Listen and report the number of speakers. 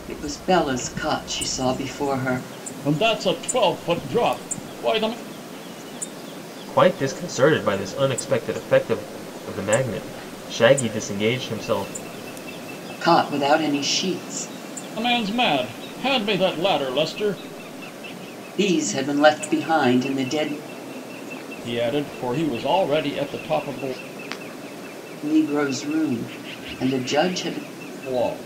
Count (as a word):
three